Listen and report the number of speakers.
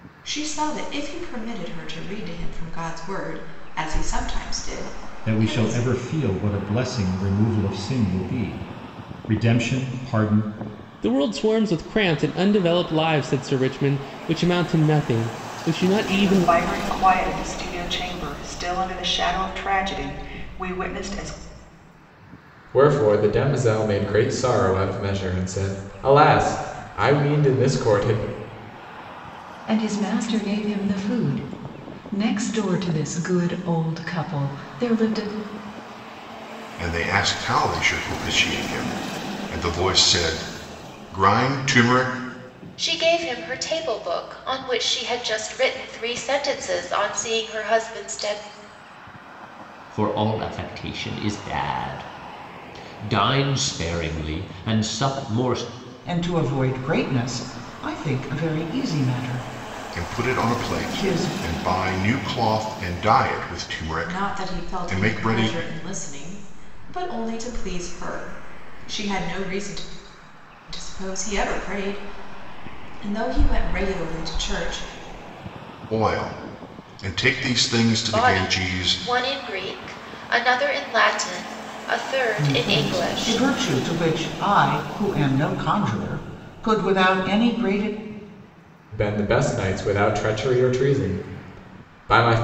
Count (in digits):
10